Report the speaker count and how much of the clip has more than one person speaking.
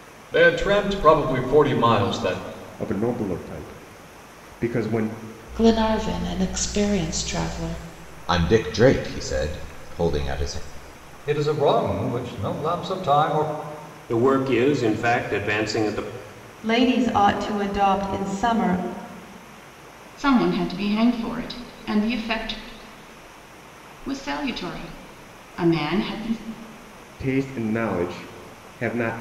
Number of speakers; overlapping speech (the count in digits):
8, no overlap